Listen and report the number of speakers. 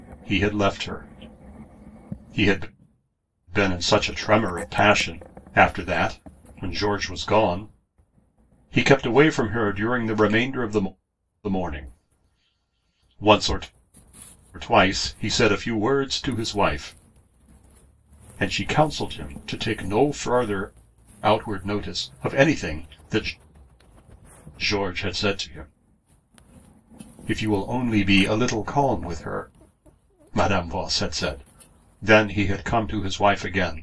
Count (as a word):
one